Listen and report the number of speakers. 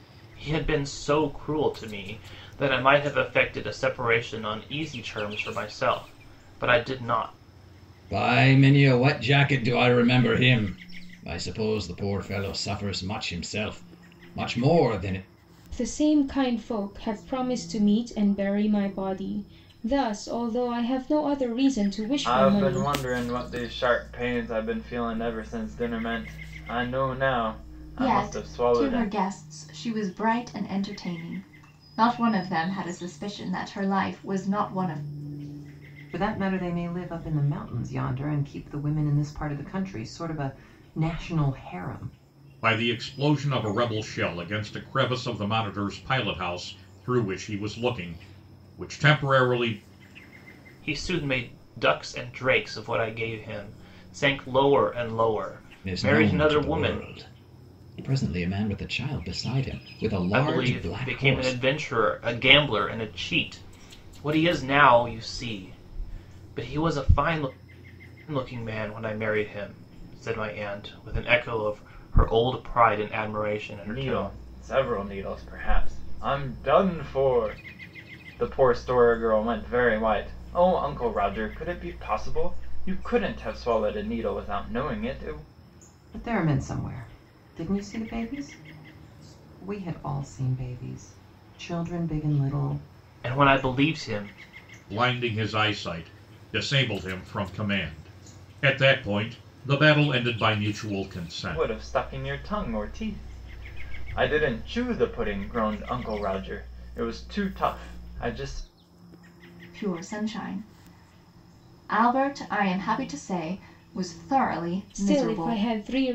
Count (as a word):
seven